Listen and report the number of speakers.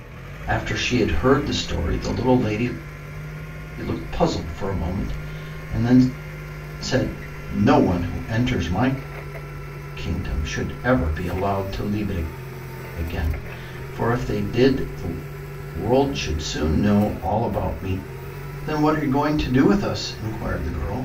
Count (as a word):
one